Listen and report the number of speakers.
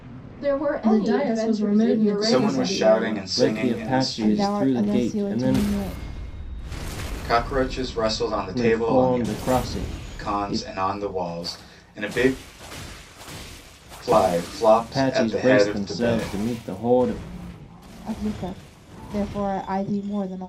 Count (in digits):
5